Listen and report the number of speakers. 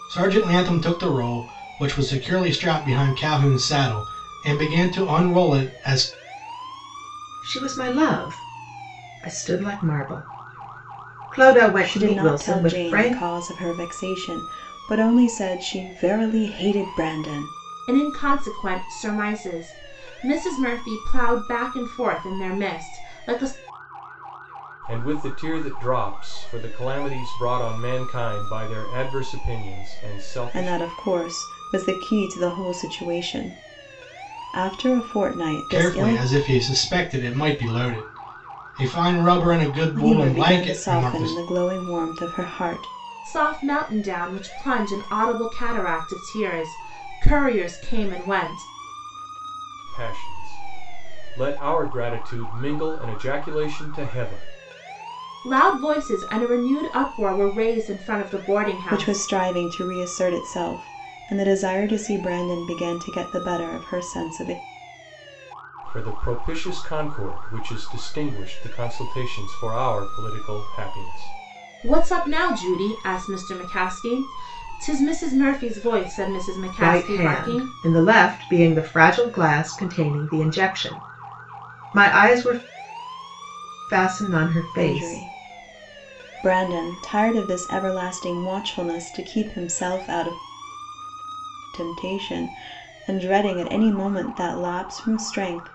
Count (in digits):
5